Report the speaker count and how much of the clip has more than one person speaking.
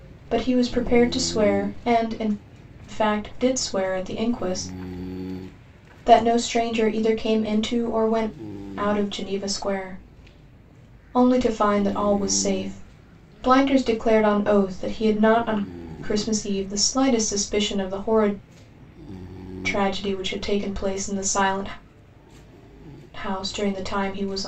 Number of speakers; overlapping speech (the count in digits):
1, no overlap